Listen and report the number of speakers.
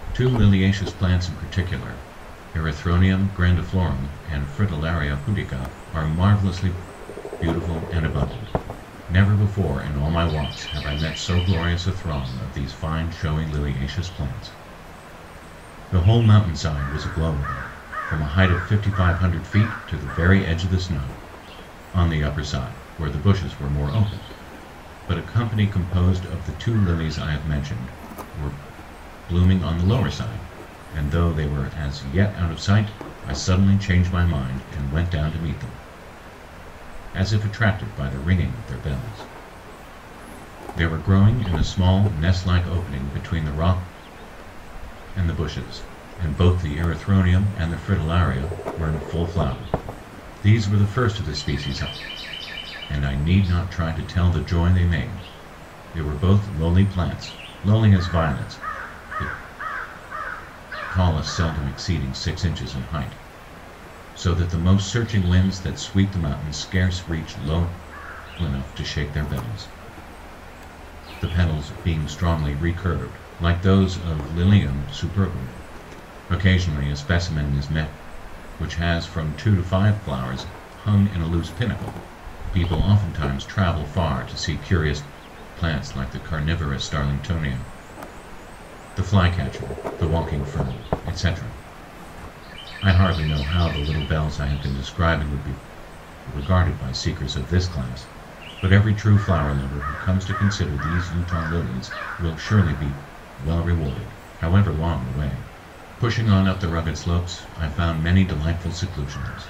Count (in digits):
1